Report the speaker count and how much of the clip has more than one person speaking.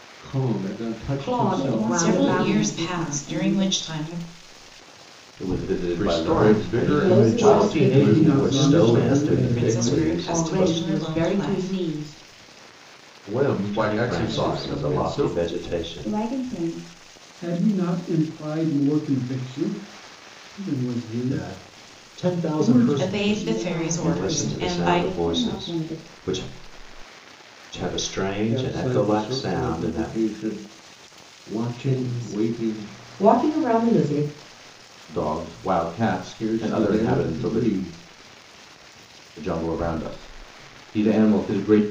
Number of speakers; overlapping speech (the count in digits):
10, about 48%